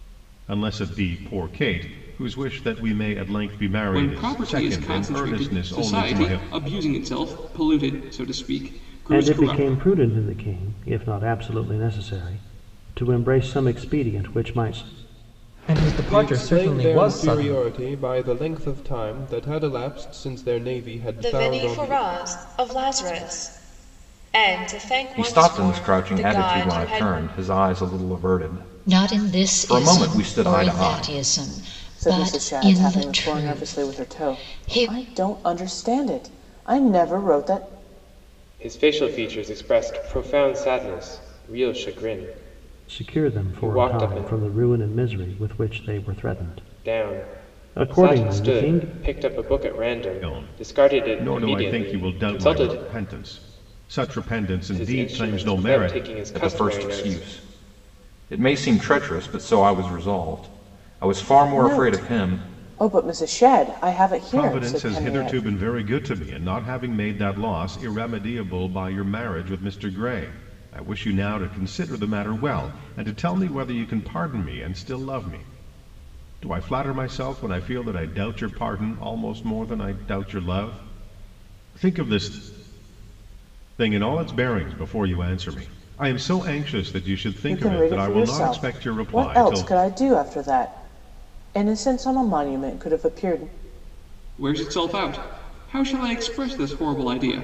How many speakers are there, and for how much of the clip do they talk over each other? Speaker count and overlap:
10, about 27%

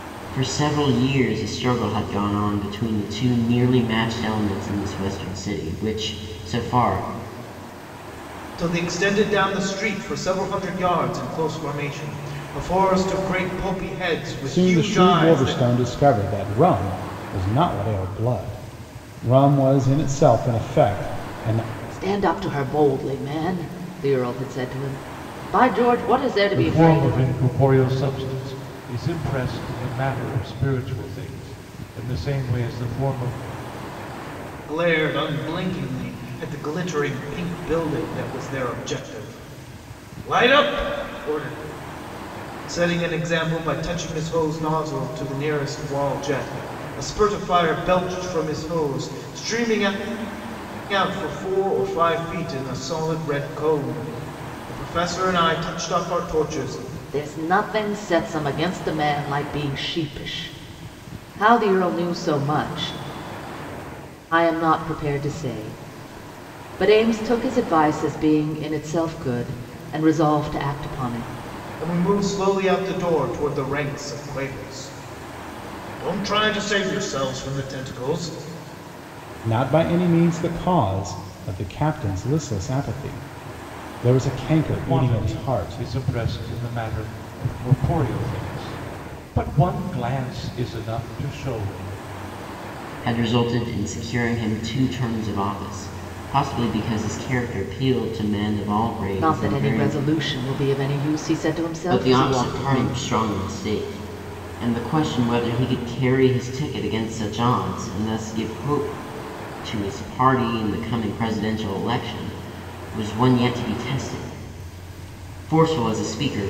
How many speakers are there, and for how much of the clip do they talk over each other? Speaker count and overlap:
5, about 5%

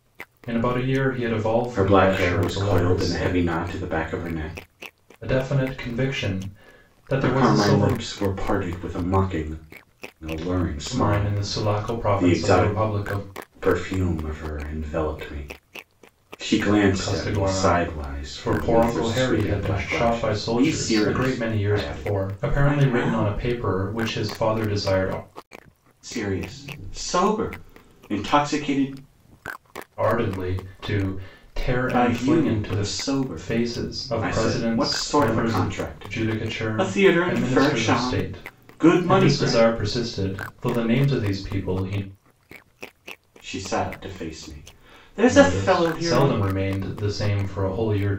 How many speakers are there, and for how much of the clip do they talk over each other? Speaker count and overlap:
2, about 38%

